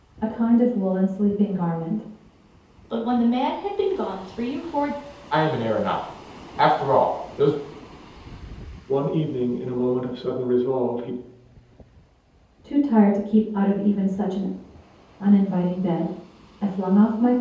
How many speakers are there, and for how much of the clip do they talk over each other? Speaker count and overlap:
four, no overlap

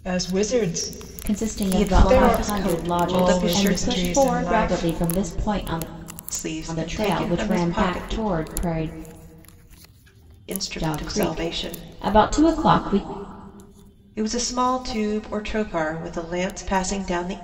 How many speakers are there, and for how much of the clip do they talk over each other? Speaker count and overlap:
three, about 37%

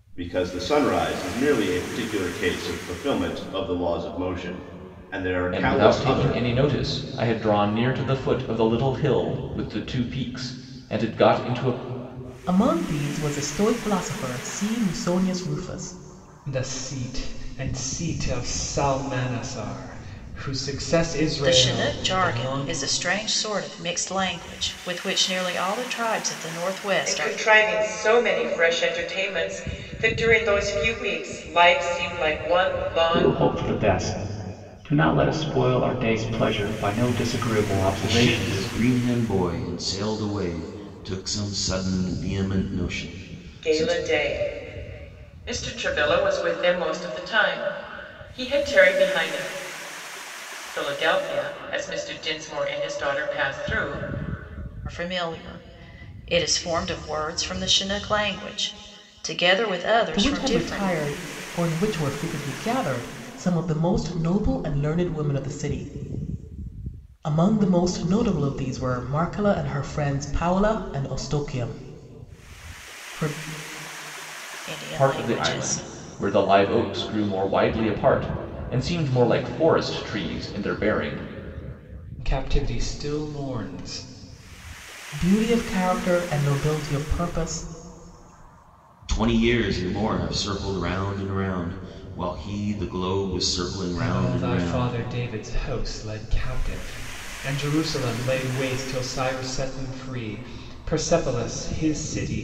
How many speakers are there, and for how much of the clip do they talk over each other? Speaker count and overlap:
eight, about 7%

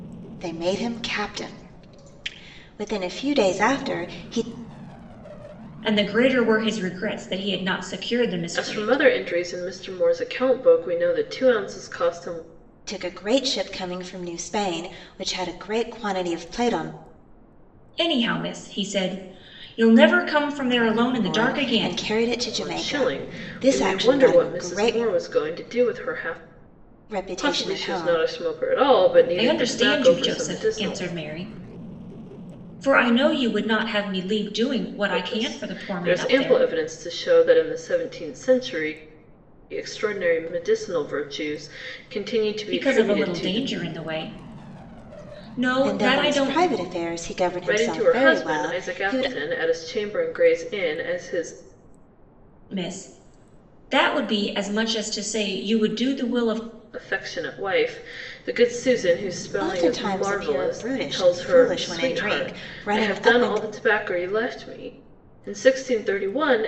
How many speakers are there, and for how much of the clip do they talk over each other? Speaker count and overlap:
three, about 24%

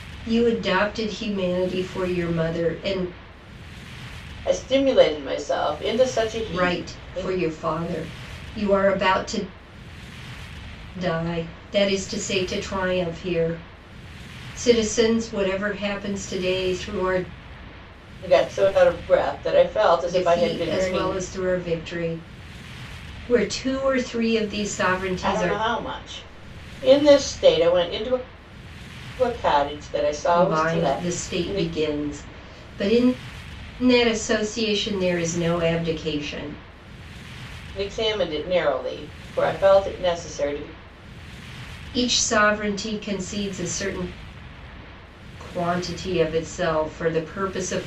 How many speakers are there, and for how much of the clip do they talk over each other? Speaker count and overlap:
two, about 8%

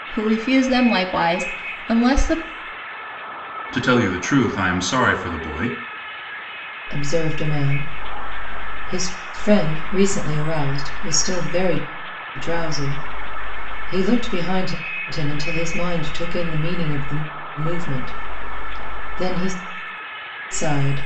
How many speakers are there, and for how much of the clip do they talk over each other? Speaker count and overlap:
three, no overlap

